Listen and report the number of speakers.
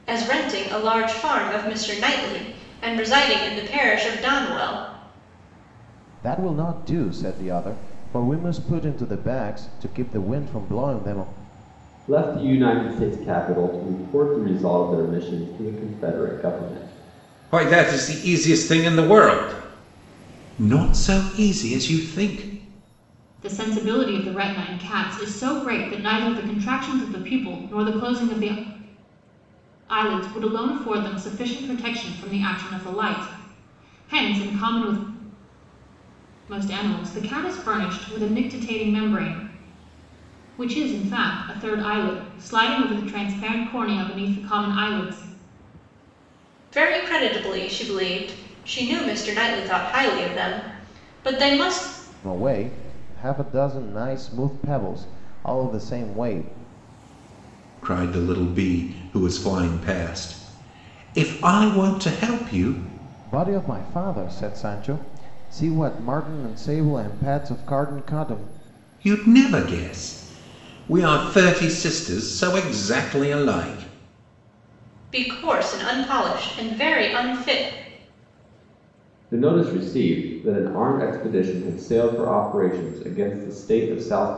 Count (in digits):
5